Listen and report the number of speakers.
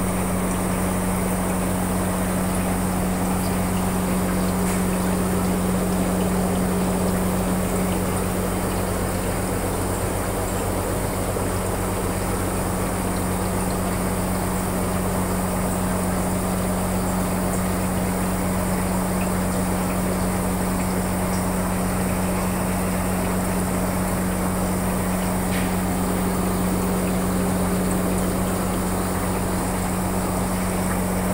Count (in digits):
0